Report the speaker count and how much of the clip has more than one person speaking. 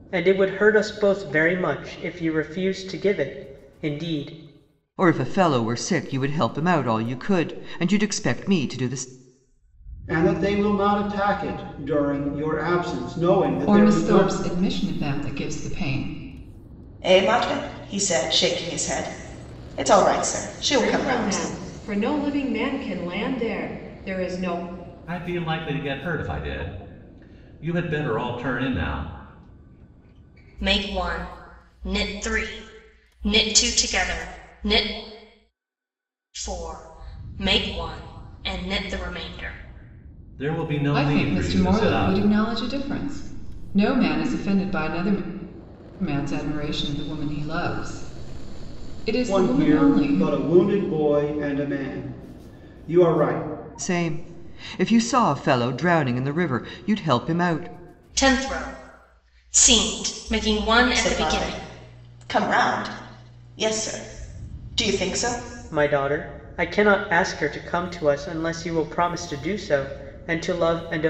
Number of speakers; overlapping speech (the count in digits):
8, about 6%